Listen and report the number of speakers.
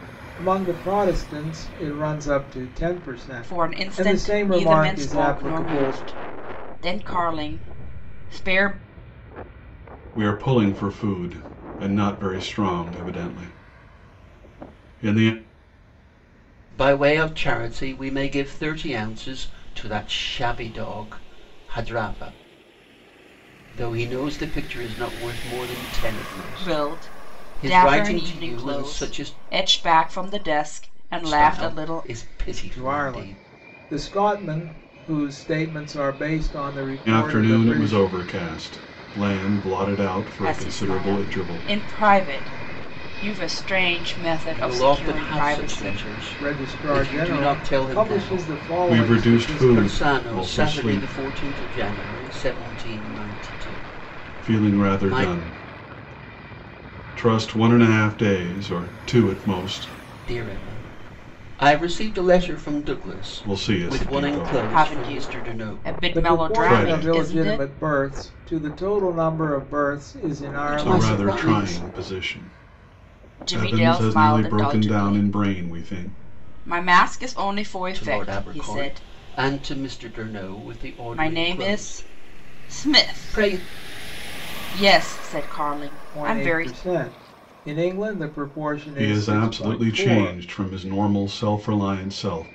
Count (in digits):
4